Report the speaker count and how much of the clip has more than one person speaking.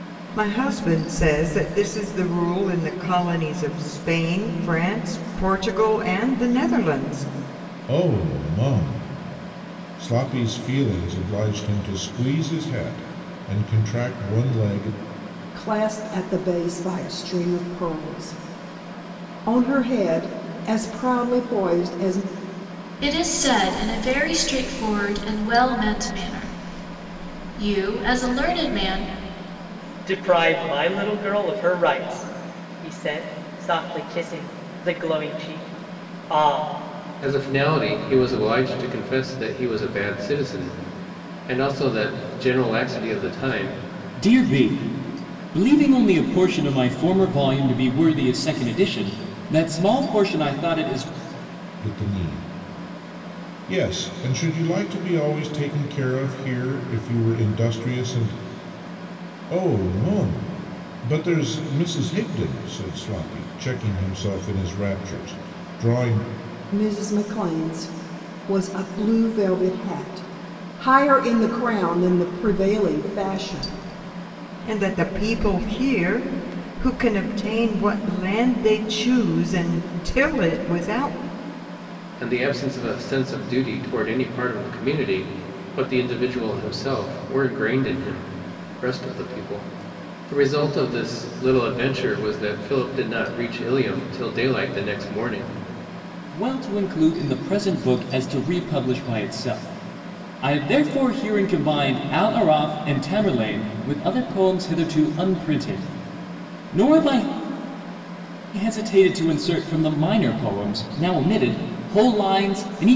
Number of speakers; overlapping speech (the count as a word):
seven, no overlap